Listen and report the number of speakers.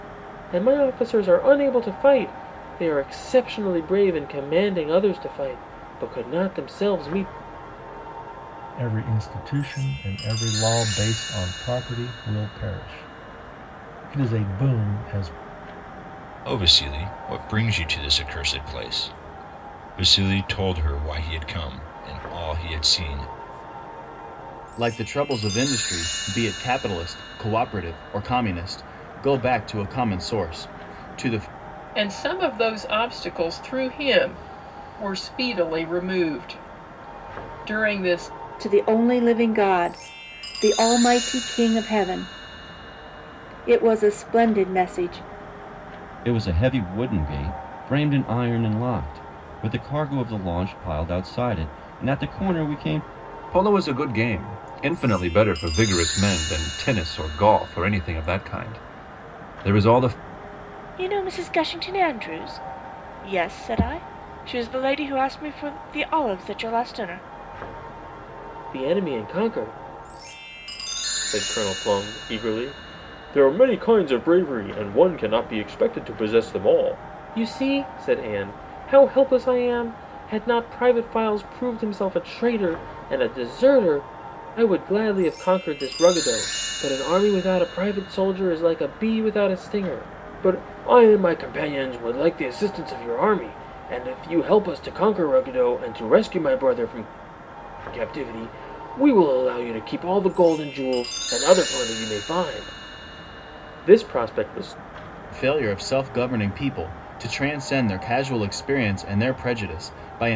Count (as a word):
nine